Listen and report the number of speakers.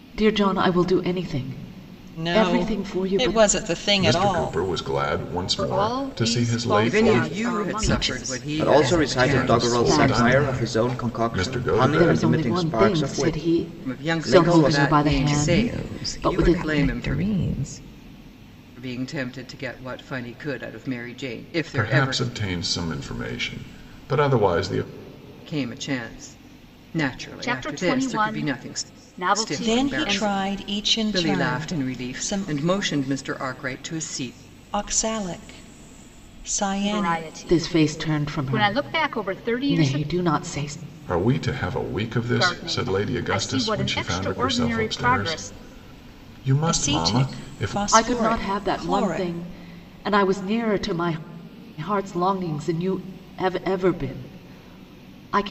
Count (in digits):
7